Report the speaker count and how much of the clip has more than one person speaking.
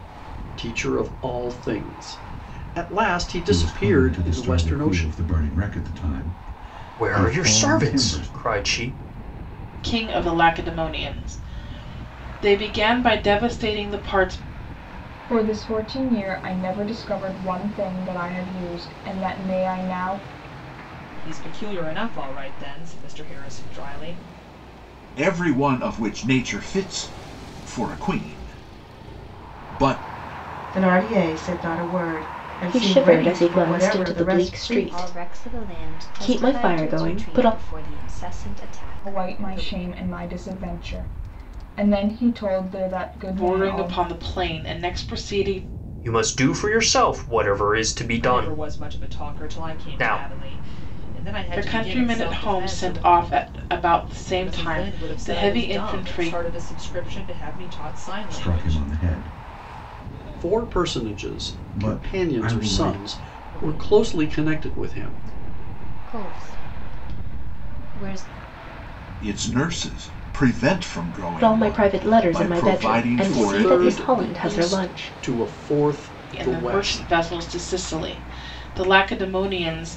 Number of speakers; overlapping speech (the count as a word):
ten, about 31%